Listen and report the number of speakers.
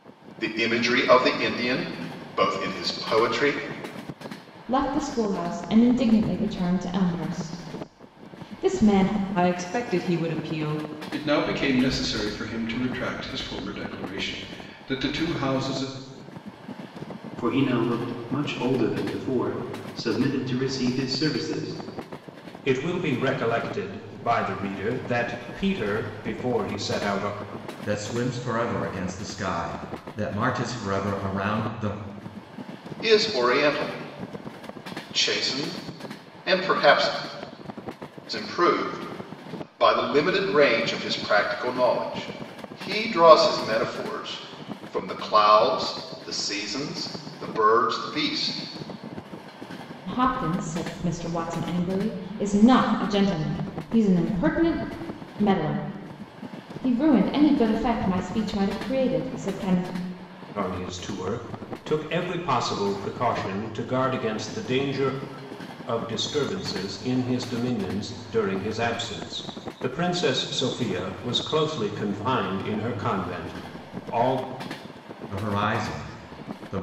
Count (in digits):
7